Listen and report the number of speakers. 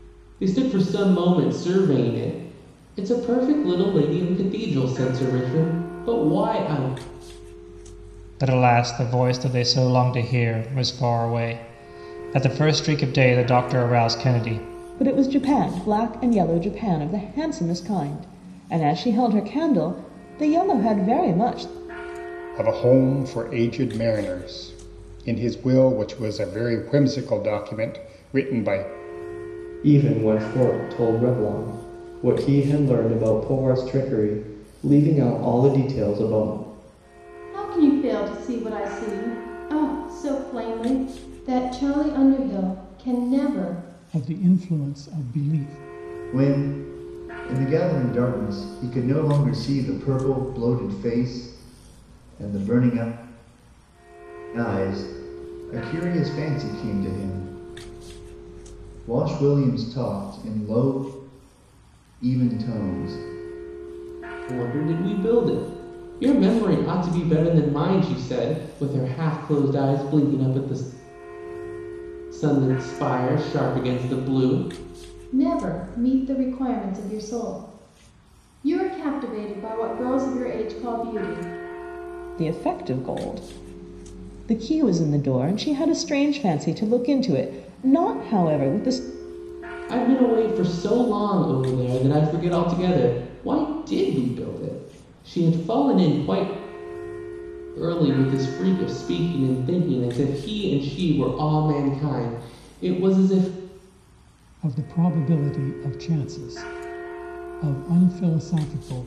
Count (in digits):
8